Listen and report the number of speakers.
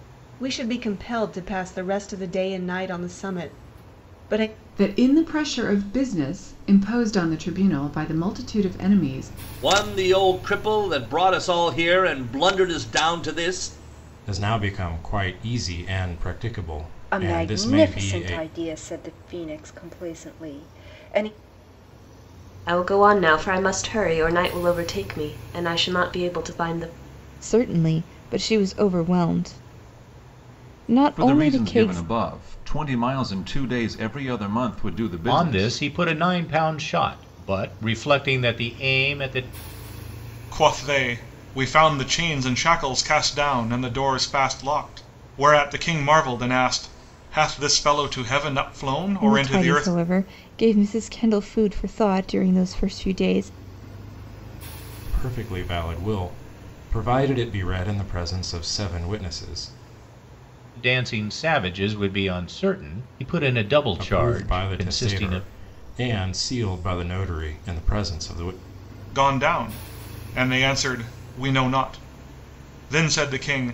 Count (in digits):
10